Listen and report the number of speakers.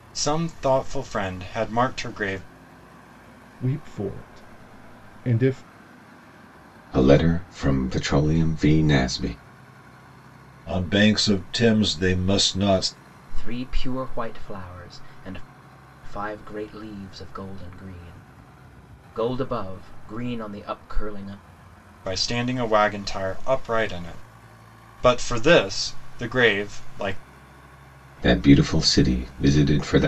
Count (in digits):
5